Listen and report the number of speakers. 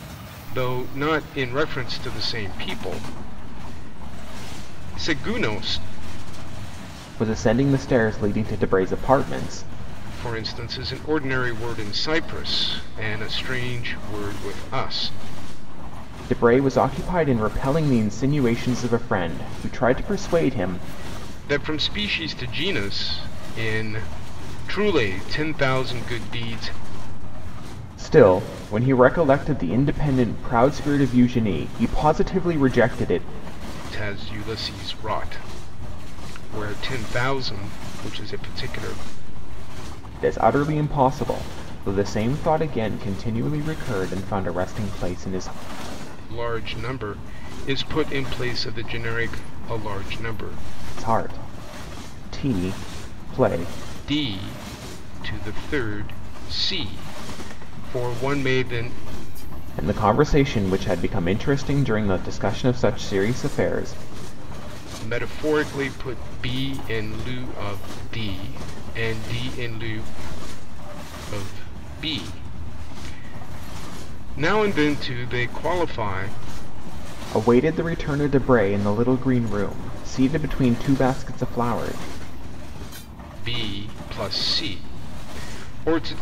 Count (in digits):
2